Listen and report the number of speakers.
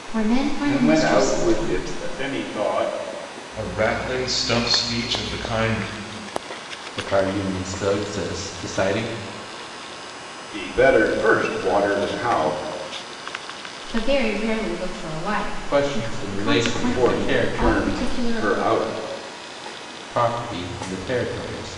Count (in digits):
4